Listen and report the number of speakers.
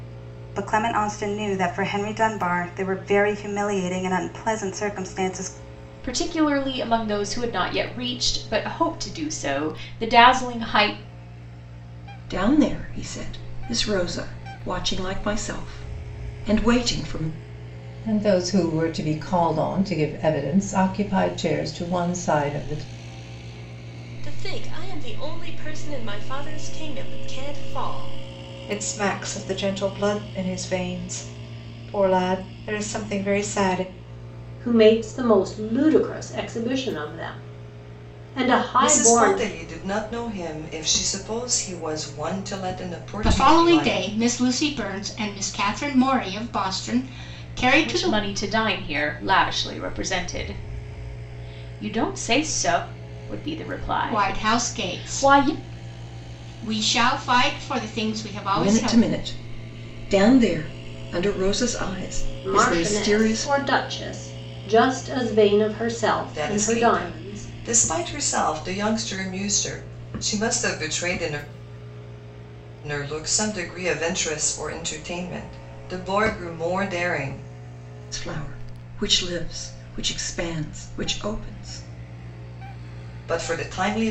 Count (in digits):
9